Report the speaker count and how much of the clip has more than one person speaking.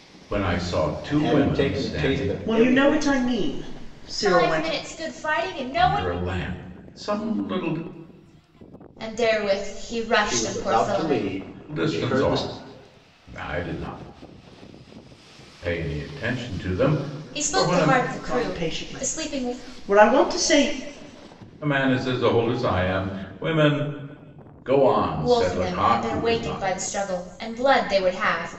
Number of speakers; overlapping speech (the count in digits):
4, about 30%